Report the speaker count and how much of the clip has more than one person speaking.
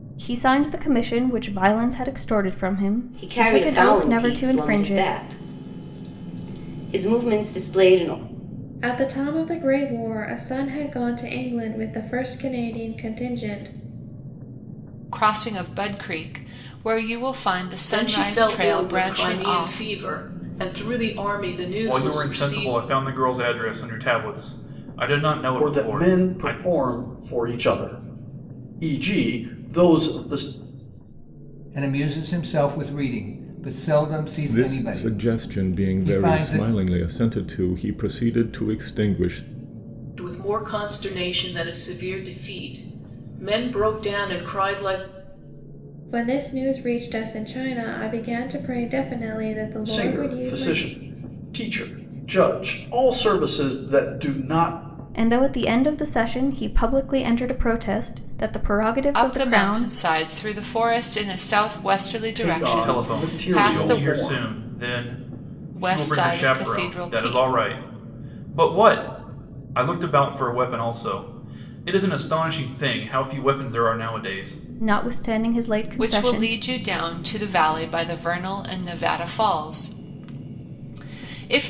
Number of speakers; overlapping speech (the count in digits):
9, about 18%